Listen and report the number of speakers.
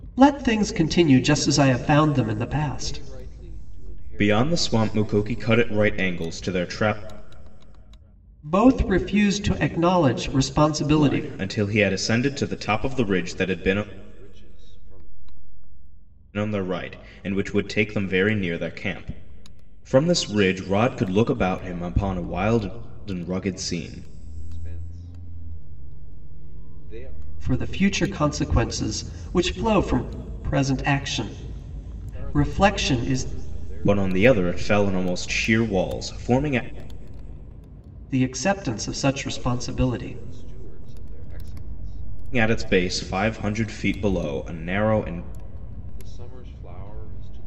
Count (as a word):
three